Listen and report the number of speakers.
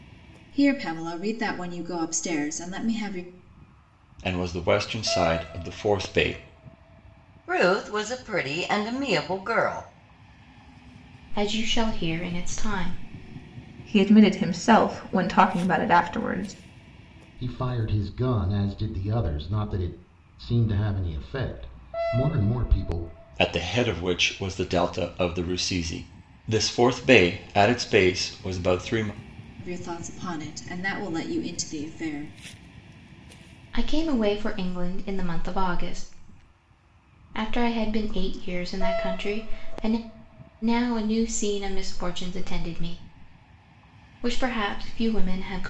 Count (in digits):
6